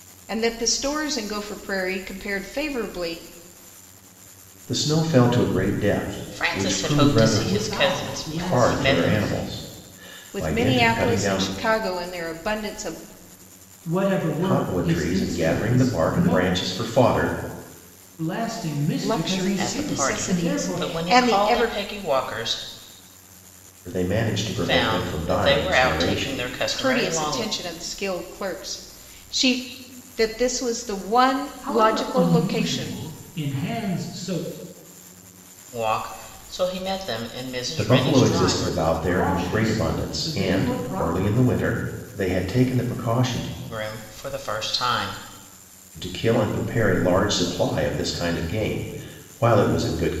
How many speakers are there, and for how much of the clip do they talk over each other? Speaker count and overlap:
four, about 34%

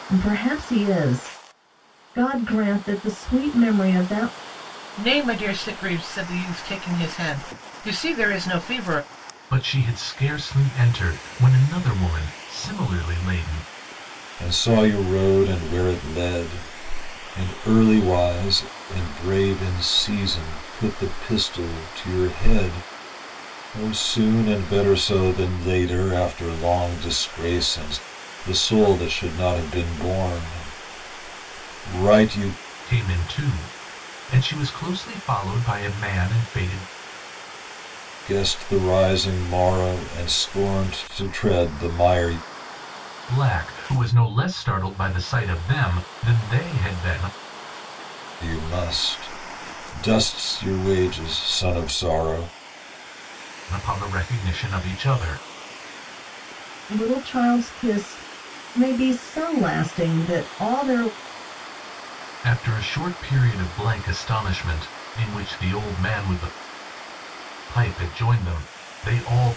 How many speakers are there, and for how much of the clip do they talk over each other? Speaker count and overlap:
four, no overlap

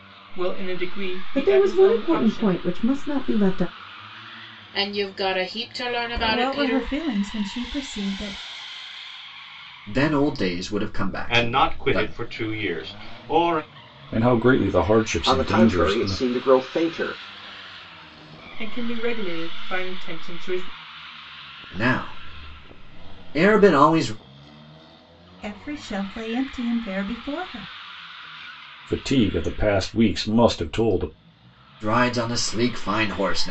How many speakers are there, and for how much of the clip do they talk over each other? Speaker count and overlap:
eight, about 12%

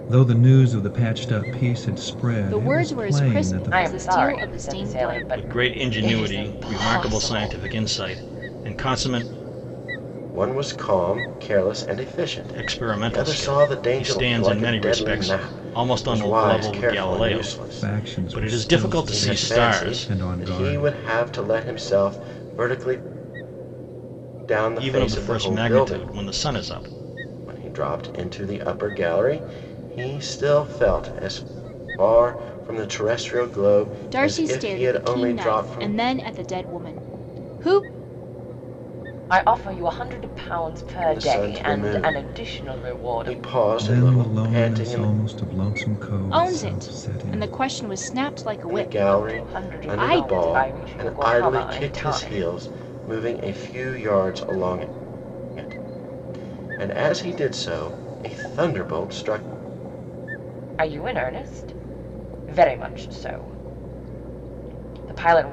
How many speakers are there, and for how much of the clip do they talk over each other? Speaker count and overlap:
five, about 38%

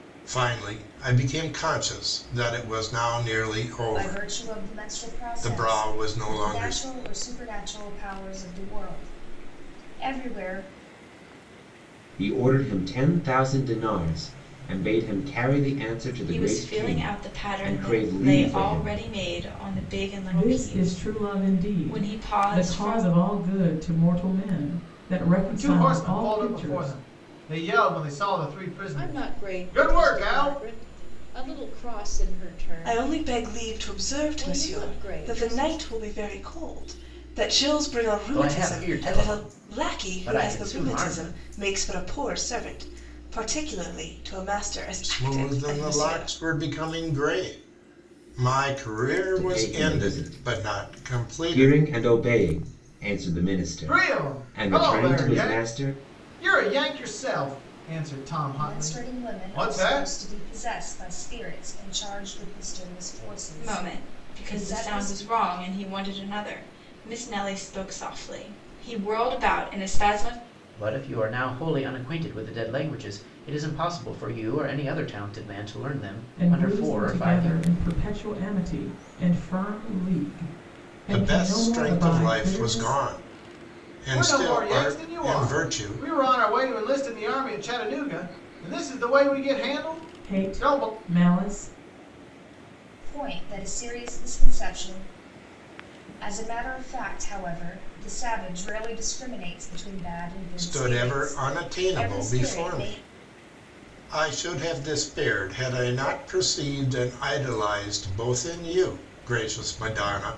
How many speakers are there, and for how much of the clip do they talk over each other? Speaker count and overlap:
nine, about 32%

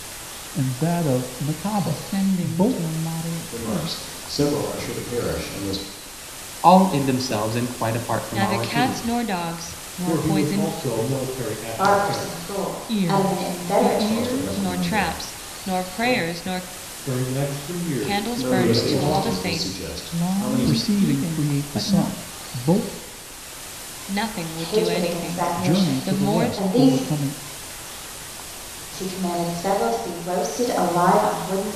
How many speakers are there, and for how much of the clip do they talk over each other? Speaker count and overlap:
seven, about 43%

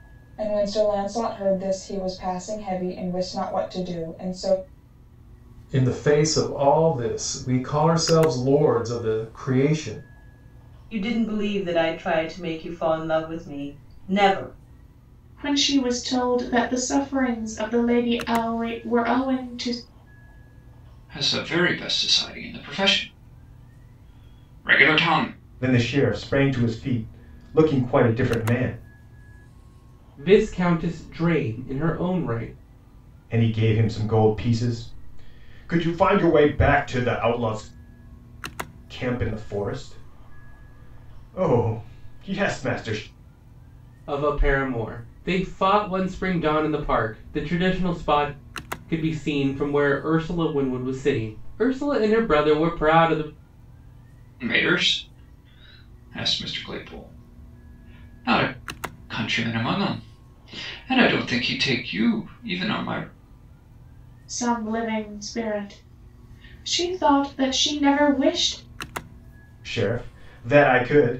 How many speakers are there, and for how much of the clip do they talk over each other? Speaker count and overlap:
seven, no overlap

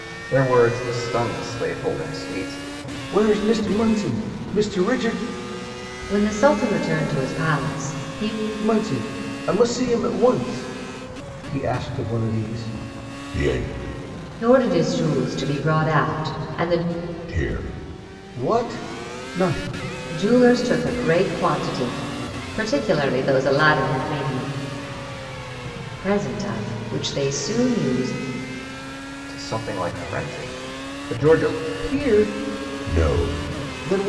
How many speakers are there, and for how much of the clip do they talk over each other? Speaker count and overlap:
three, no overlap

